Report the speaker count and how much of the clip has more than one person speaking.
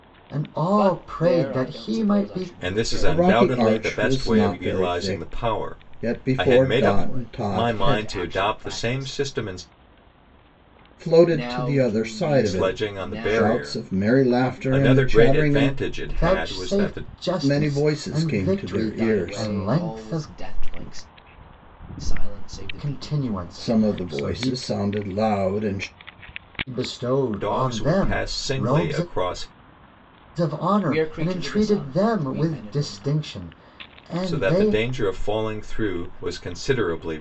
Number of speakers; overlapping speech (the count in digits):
4, about 58%